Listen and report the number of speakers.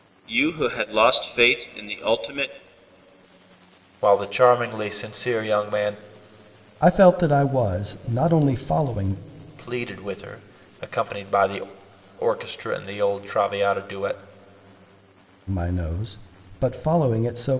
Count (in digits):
3